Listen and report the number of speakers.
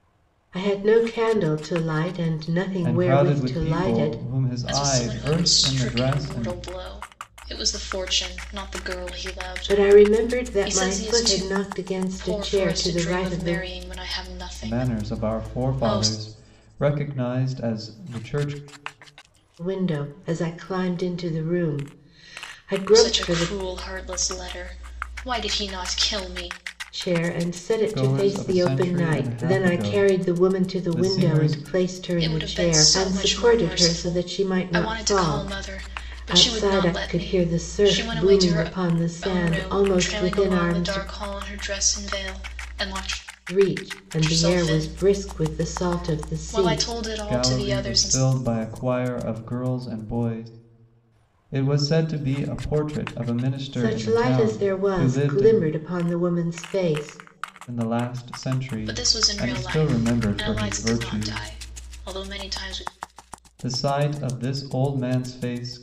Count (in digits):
3